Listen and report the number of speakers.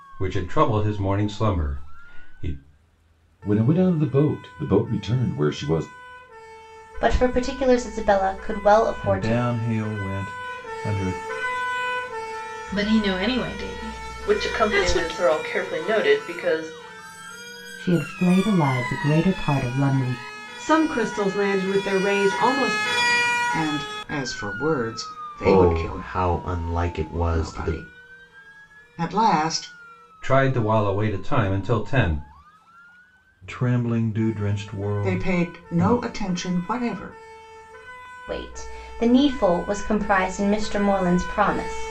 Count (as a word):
ten